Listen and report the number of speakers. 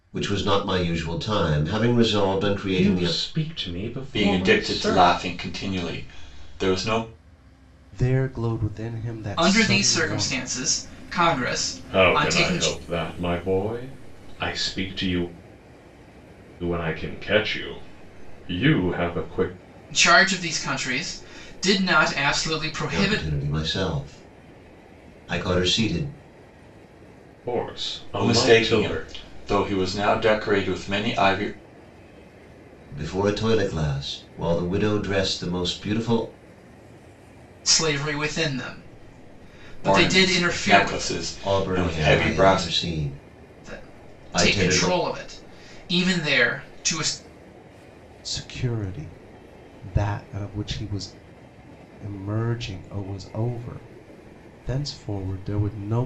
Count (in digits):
5